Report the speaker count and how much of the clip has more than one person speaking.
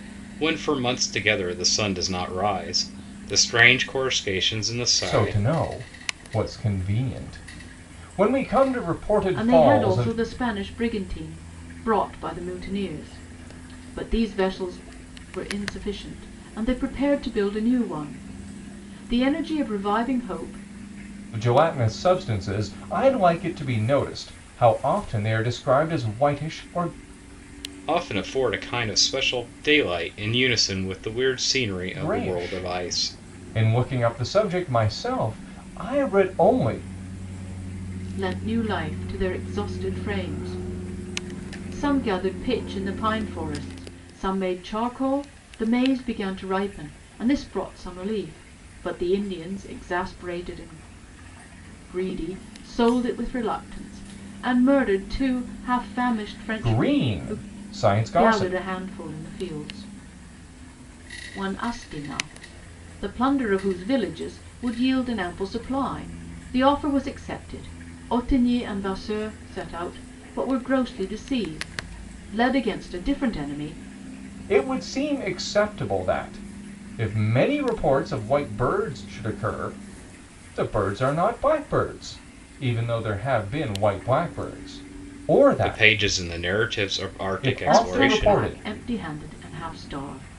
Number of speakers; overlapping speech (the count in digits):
3, about 6%